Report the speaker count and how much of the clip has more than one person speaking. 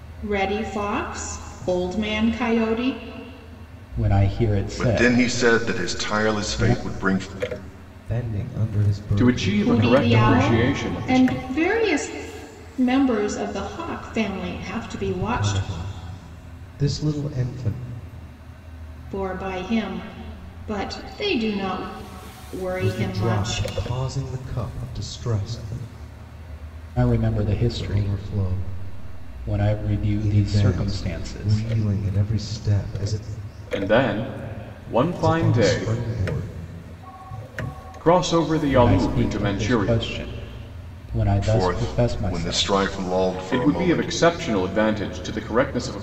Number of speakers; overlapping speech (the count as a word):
five, about 30%